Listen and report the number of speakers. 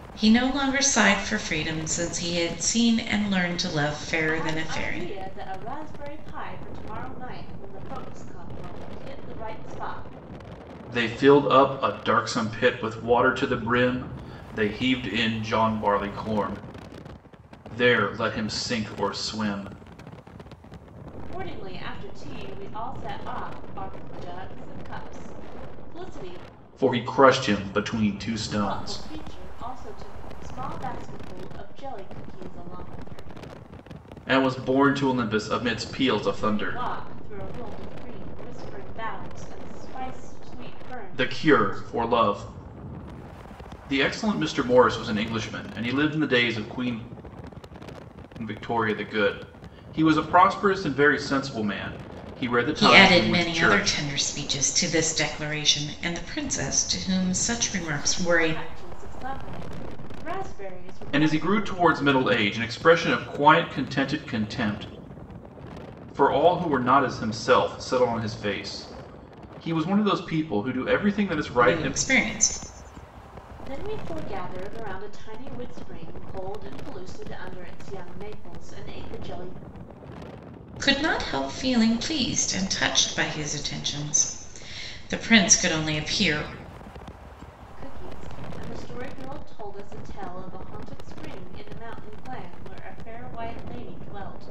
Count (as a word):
three